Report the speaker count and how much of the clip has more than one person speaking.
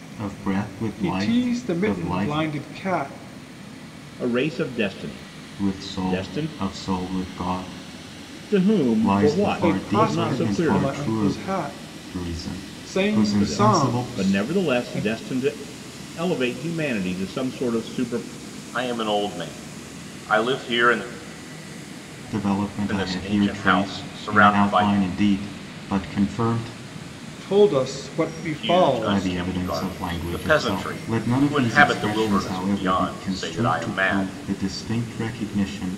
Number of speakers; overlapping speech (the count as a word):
three, about 42%